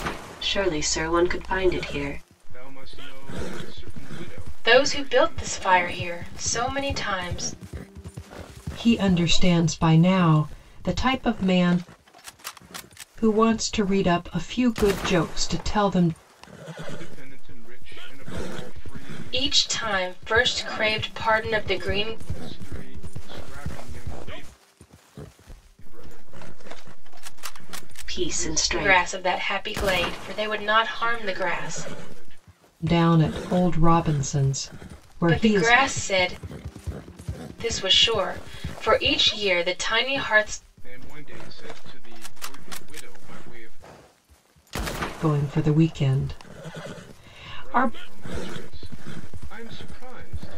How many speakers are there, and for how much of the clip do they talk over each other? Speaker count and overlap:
4, about 10%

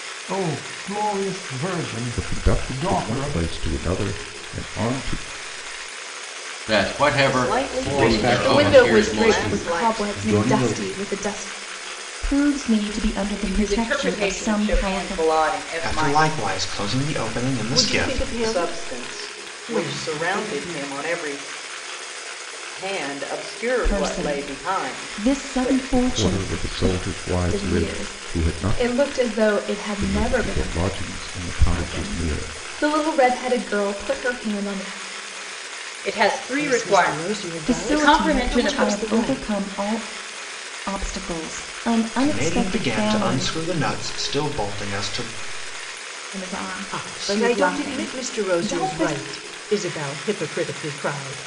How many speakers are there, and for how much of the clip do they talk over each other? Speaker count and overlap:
10, about 45%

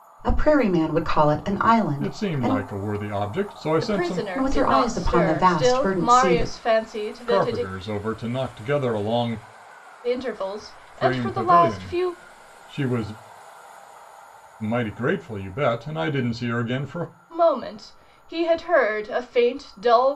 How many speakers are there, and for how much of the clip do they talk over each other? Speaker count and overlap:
3, about 26%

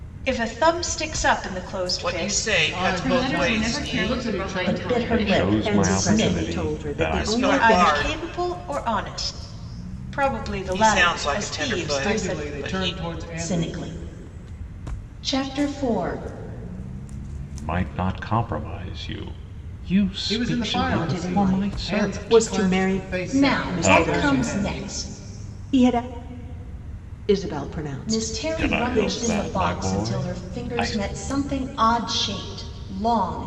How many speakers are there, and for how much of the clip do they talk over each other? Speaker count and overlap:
7, about 51%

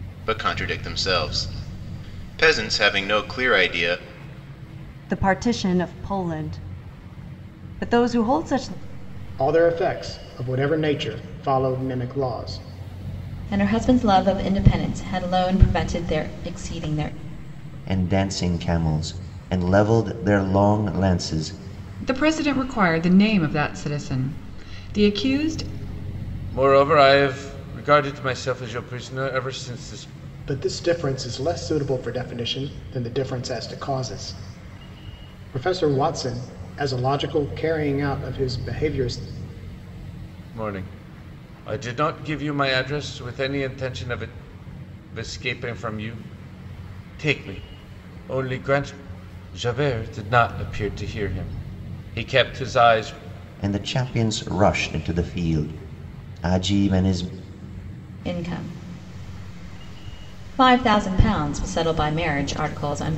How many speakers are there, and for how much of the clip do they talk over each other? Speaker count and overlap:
7, no overlap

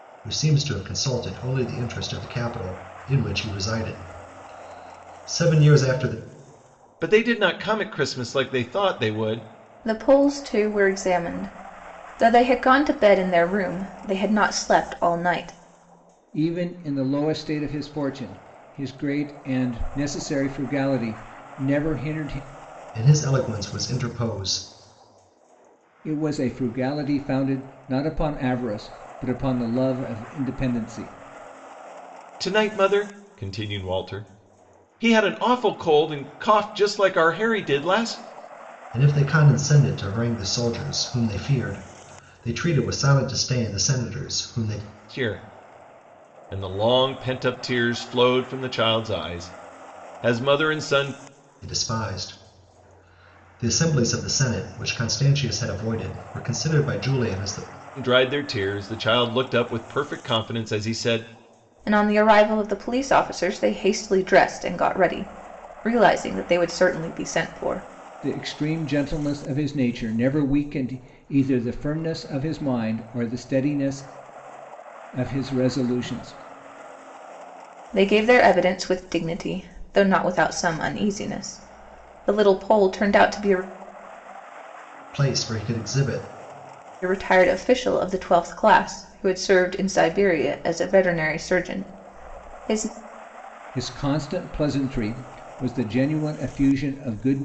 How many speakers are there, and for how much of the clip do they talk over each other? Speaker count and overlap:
4, no overlap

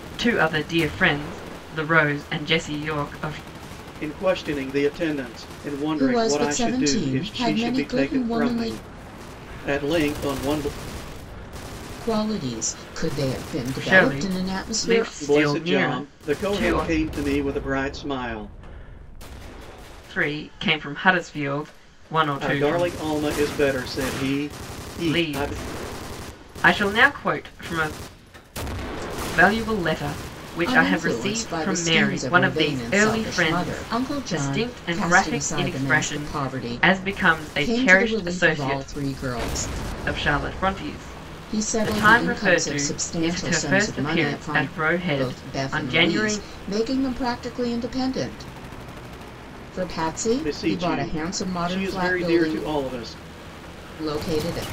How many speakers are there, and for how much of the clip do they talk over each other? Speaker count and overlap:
3, about 39%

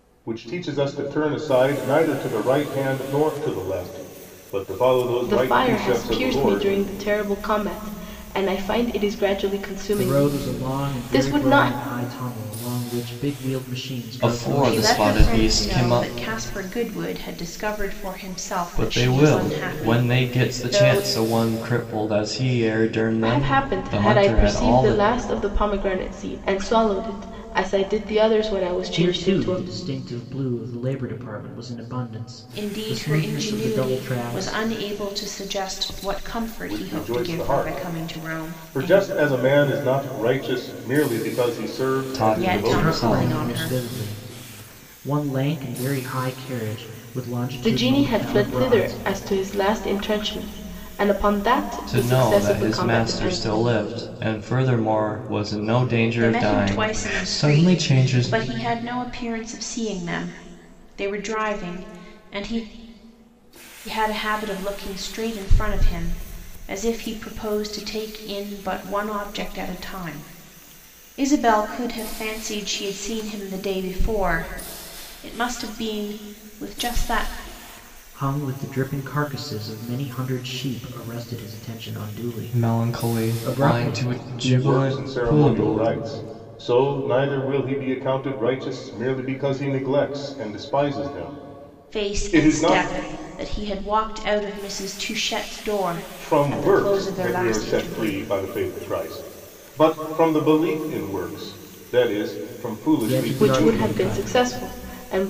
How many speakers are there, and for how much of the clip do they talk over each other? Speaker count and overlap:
5, about 28%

